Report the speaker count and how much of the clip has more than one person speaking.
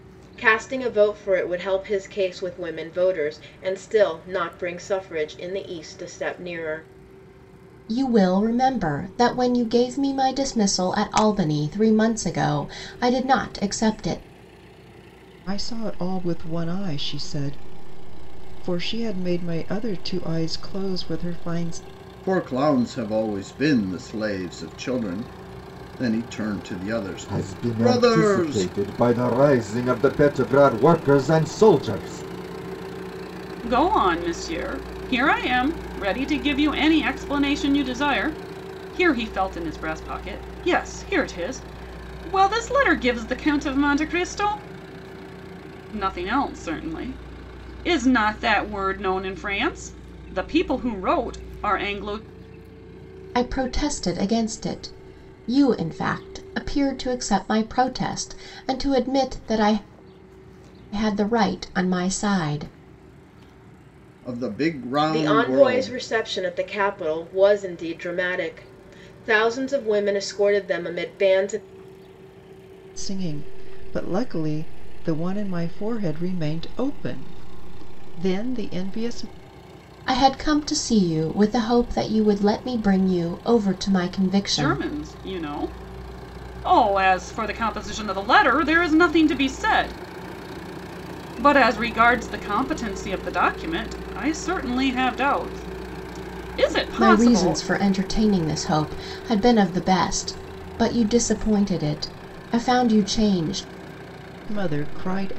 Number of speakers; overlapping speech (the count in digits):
6, about 3%